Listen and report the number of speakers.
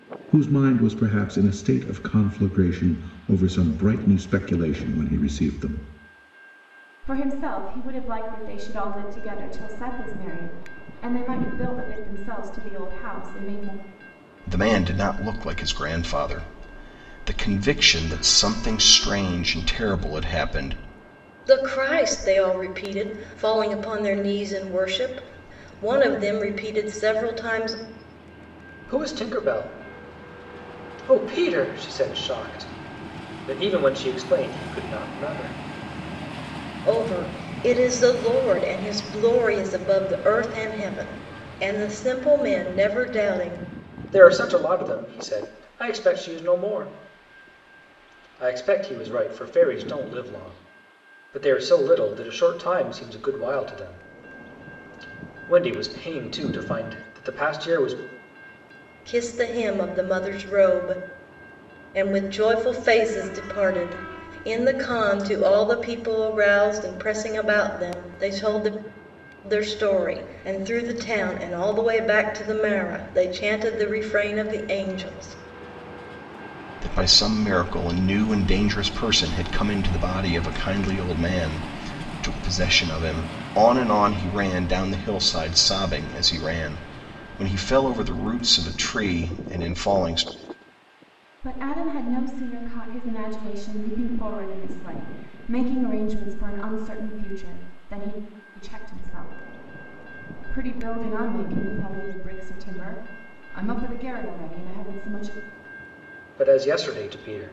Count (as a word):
five